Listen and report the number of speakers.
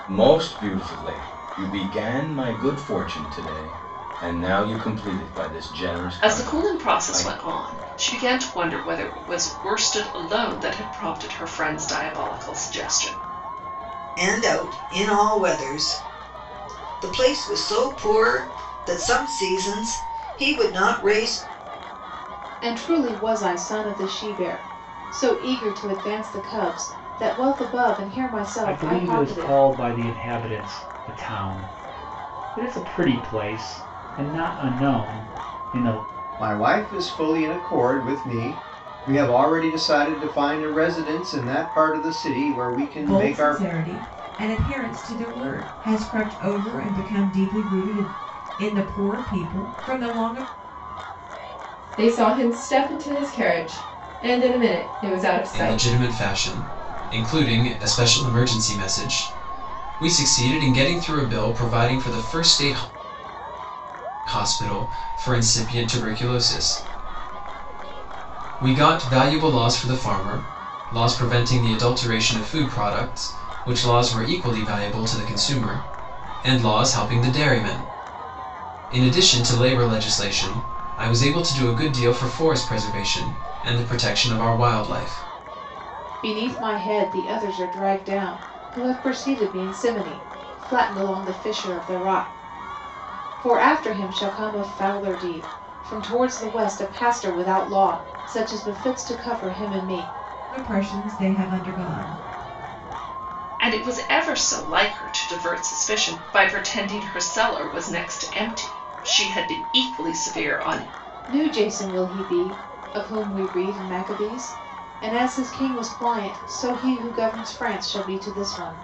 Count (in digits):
9